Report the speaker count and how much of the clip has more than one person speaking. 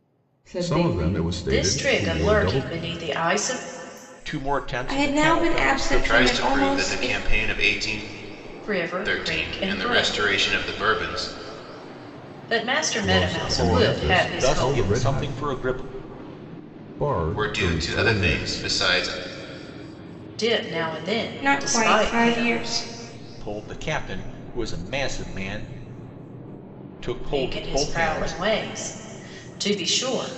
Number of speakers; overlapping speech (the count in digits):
6, about 39%